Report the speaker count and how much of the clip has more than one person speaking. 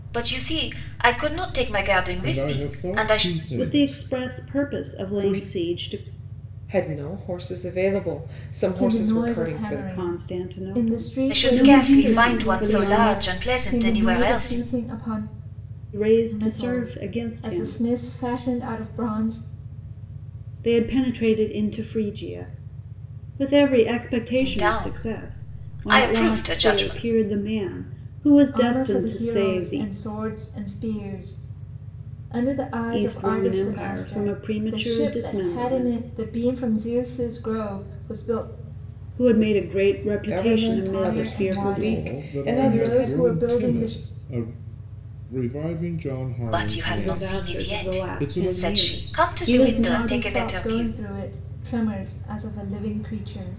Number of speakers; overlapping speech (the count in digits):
5, about 49%